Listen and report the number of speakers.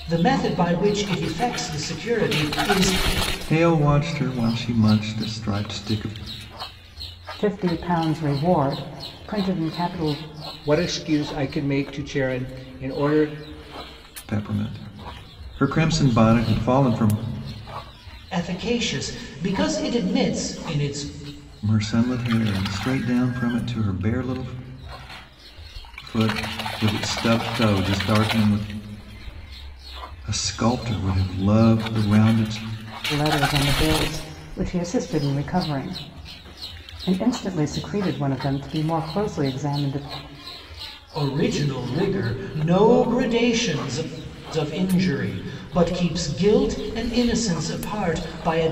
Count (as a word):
four